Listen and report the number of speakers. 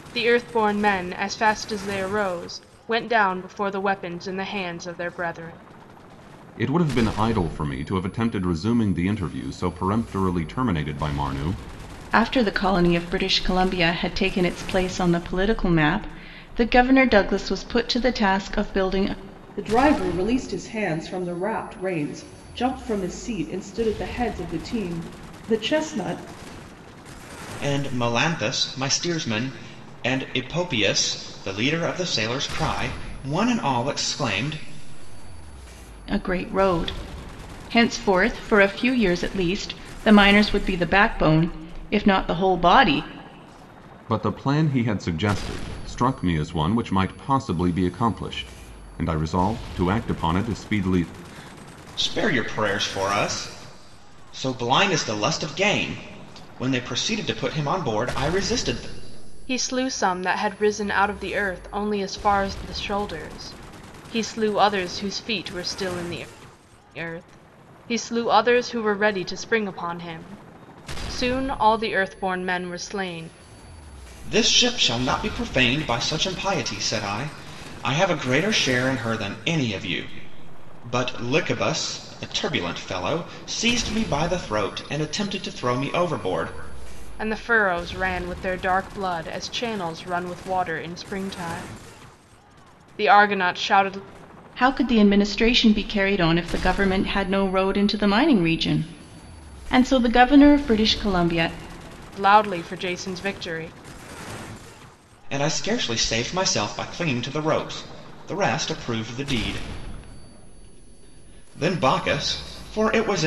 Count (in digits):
5